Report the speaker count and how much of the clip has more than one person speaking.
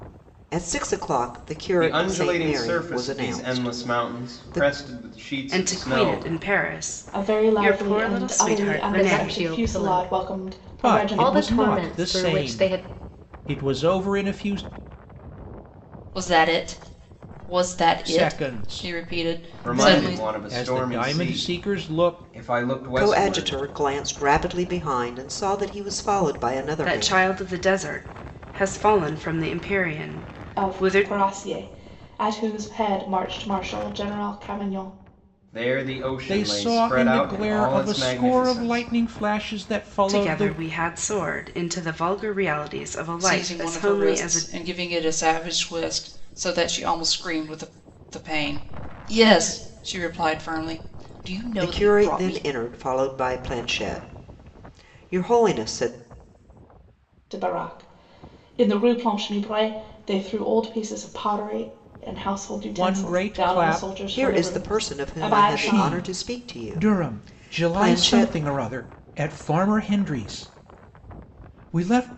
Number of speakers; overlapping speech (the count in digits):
7, about 37%